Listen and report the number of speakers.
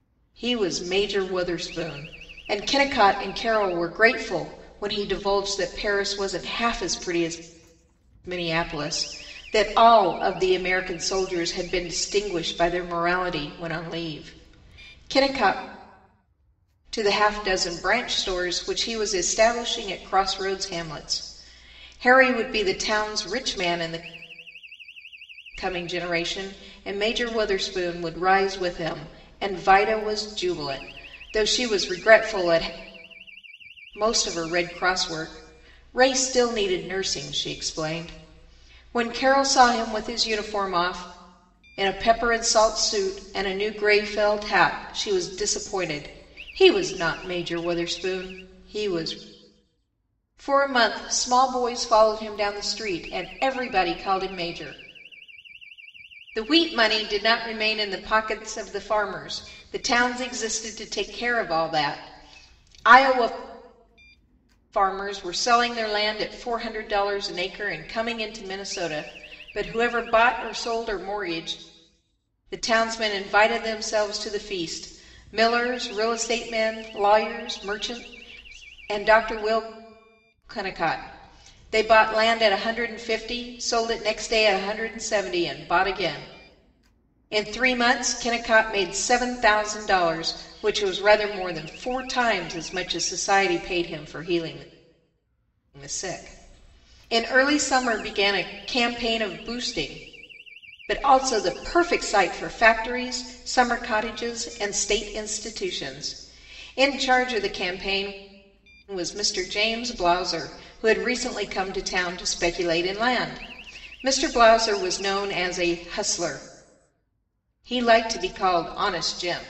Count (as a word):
one